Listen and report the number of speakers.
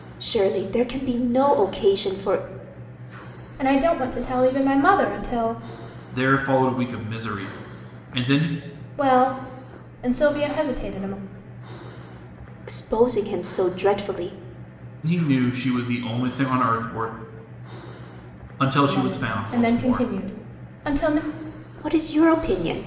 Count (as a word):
three